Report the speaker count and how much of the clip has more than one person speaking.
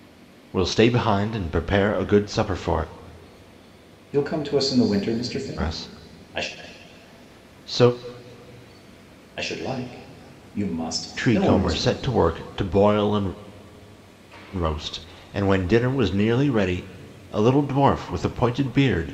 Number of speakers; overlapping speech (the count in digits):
2, about 9%